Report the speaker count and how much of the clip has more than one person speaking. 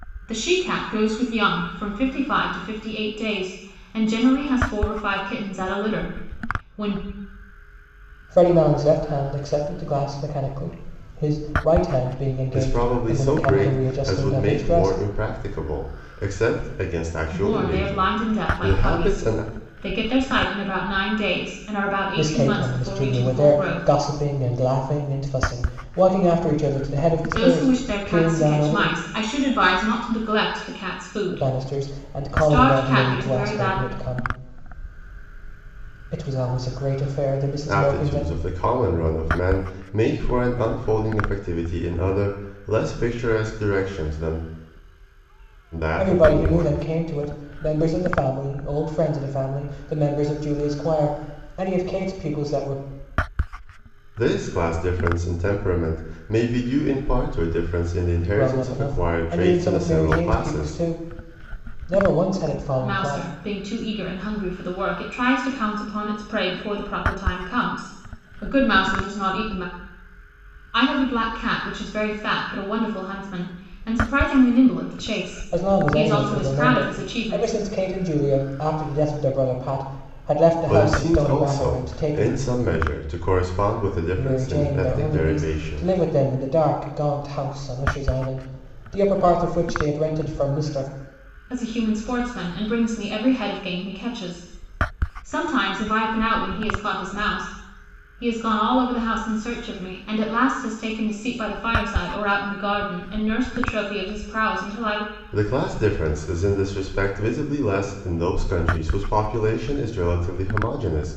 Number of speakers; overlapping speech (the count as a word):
three, about 19%